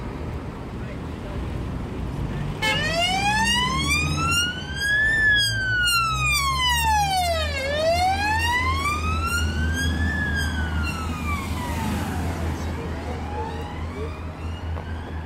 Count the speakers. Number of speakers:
0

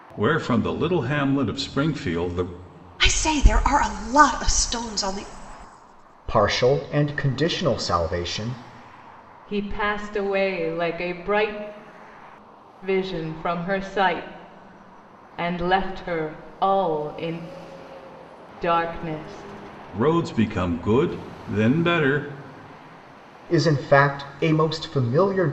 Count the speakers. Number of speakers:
4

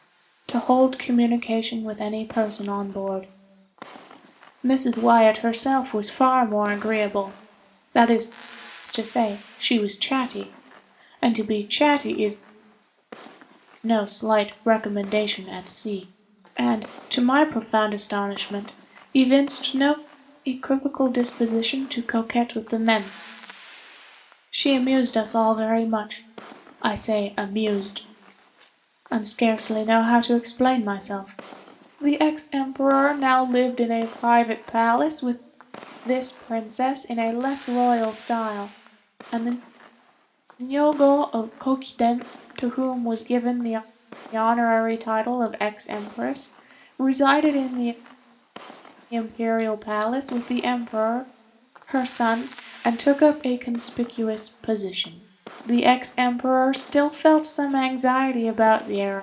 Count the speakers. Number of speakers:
1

